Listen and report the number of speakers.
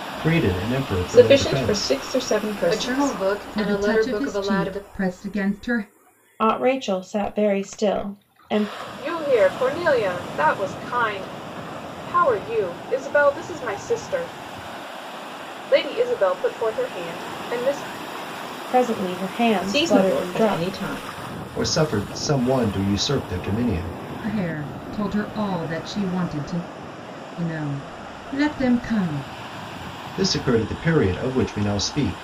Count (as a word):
six